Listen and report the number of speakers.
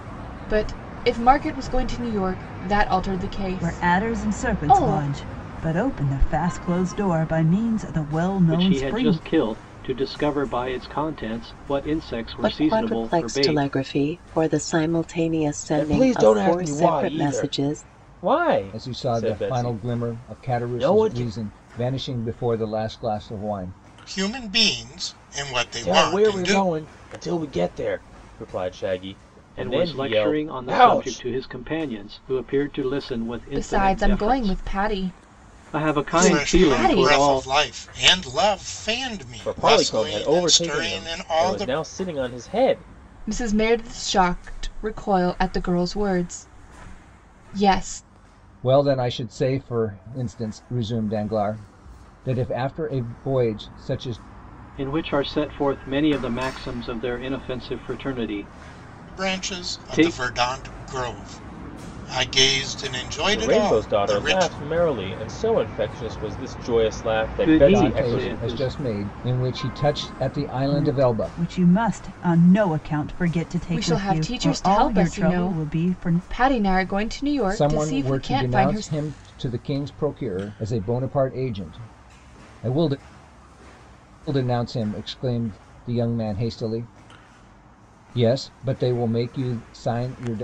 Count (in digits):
7